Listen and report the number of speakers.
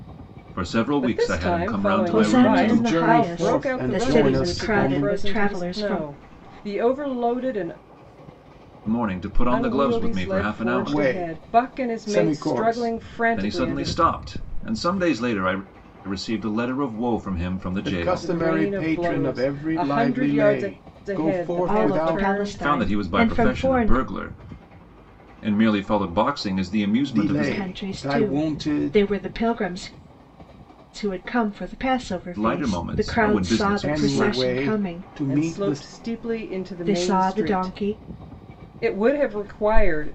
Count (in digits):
4